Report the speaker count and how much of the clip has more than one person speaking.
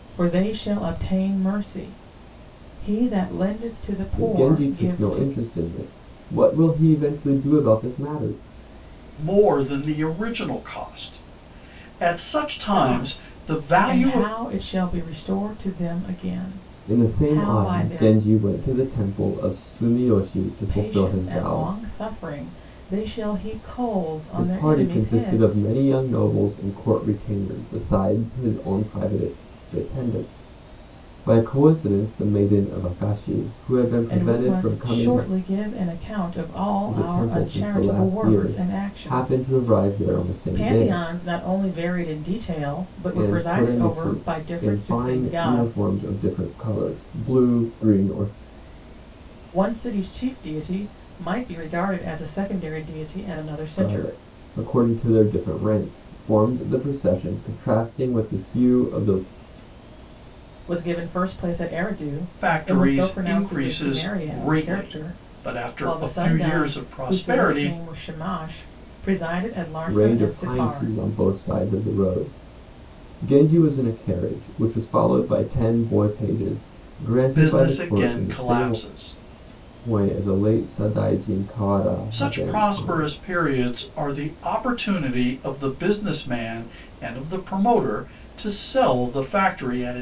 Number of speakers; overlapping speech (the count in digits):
3, about 25%